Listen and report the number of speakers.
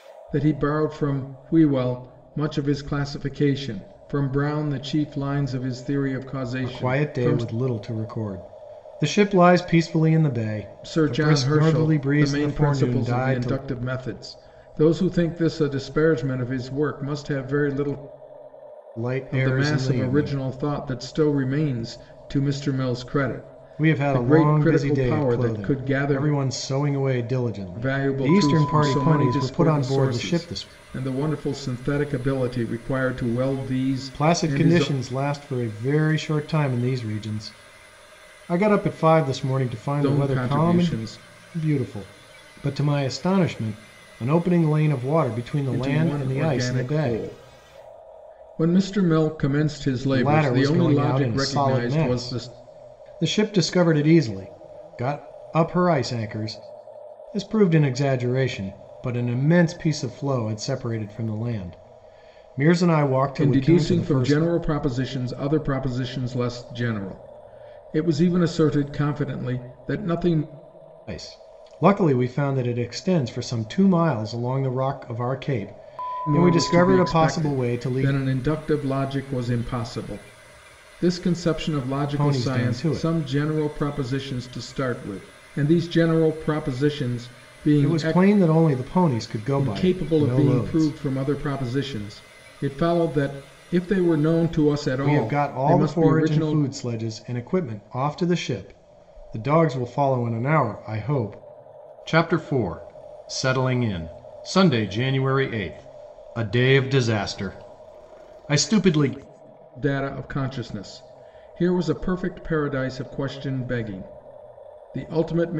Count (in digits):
2